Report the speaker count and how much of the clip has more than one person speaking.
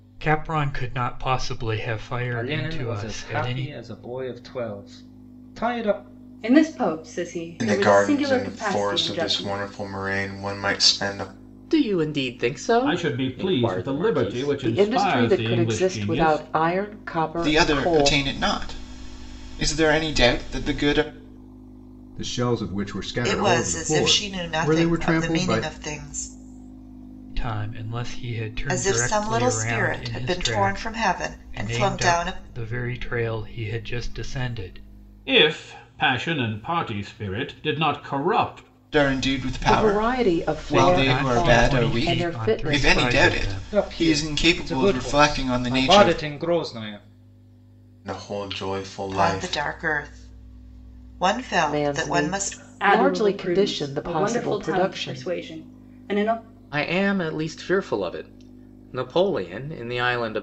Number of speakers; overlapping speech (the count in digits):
10, about 40%